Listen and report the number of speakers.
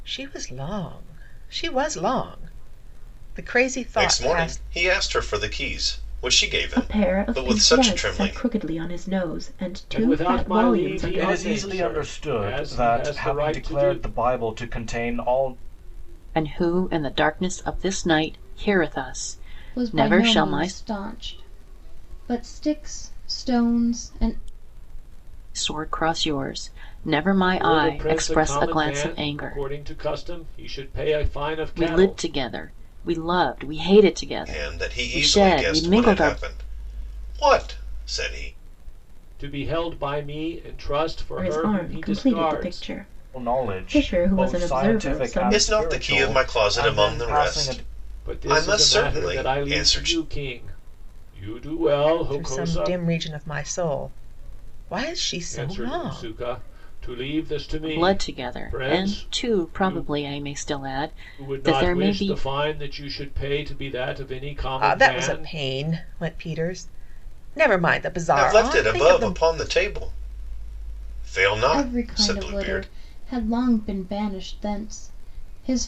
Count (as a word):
seven